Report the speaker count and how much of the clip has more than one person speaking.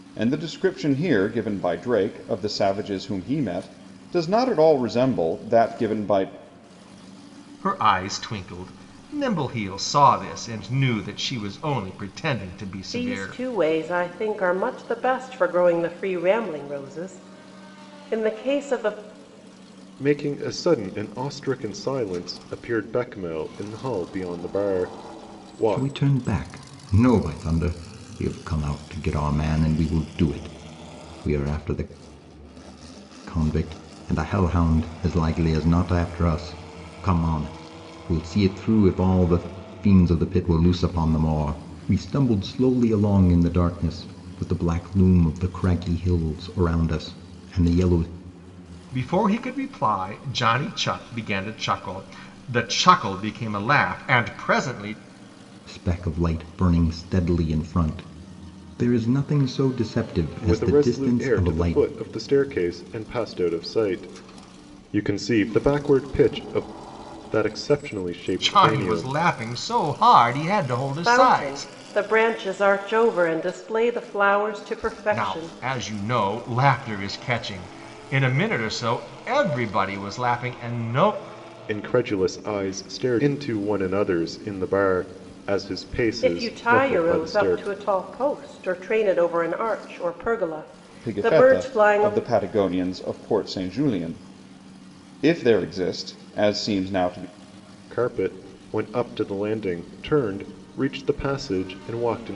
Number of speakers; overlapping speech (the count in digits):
5, about 7%